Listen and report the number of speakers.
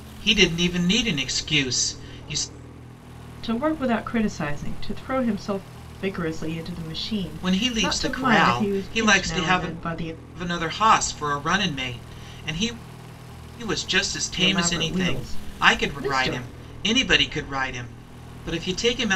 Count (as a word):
two